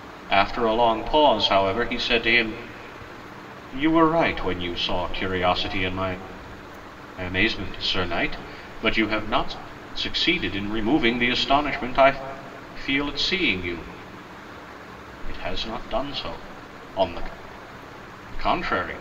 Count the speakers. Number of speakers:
one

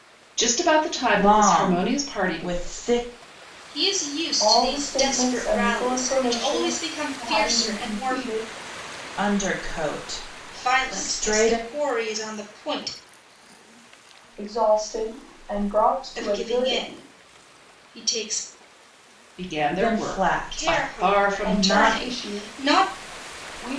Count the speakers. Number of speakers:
four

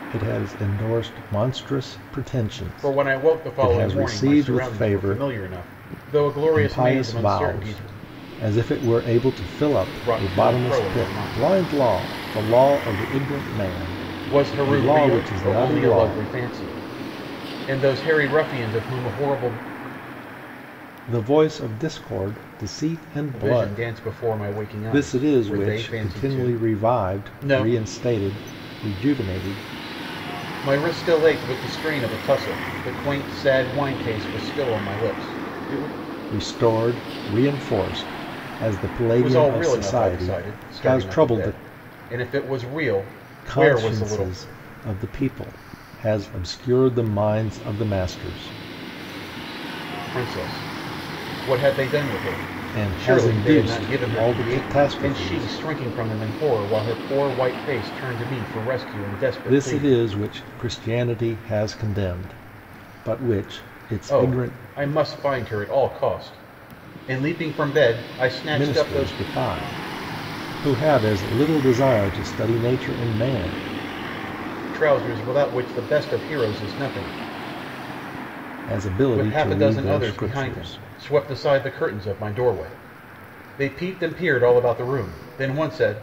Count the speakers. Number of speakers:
two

